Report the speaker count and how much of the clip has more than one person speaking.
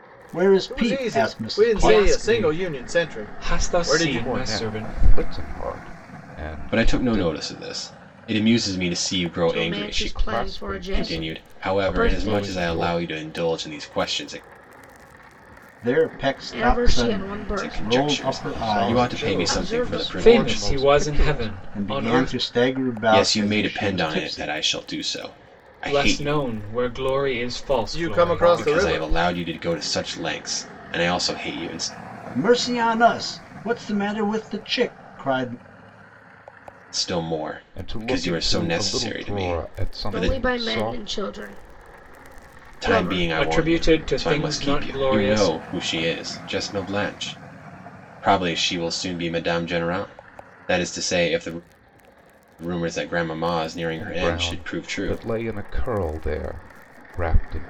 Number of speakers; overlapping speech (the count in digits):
6, about 44%